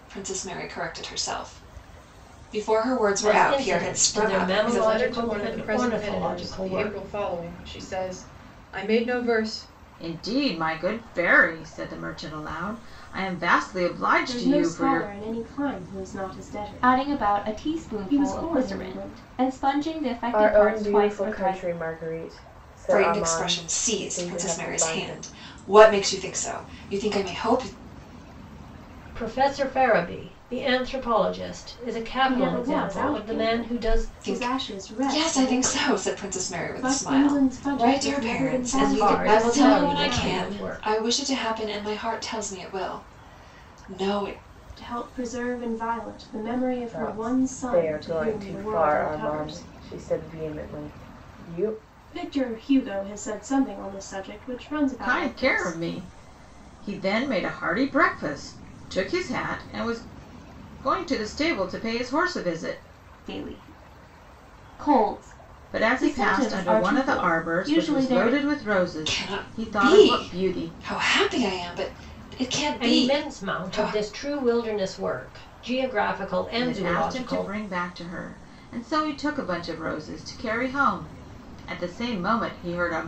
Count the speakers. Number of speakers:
seven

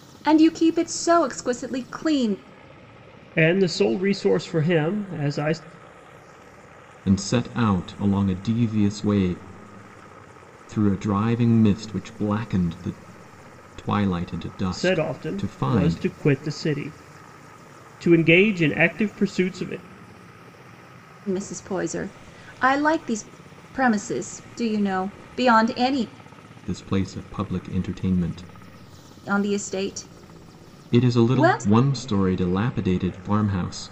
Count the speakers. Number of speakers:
three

